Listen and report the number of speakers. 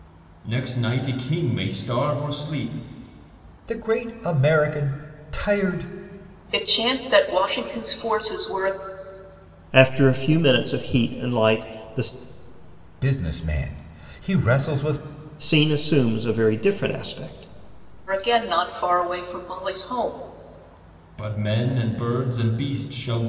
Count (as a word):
four